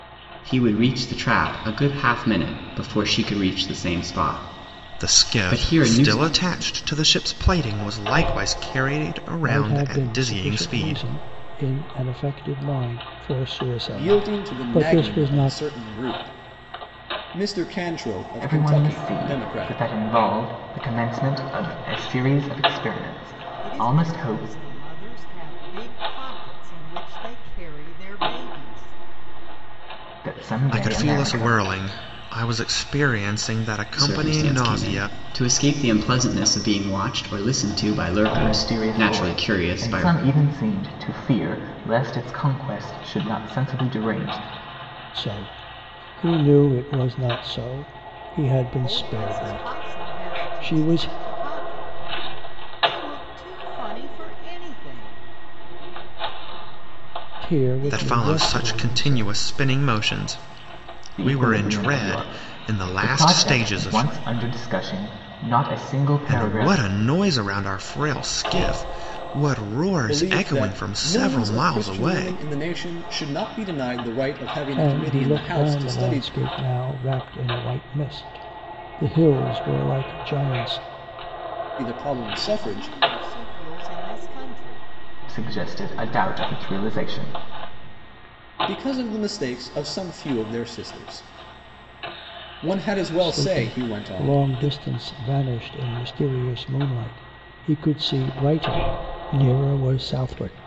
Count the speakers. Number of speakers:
6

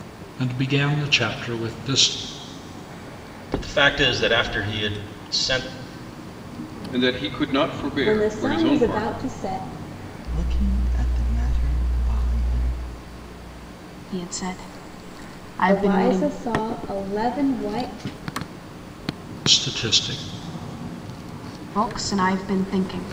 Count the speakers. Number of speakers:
6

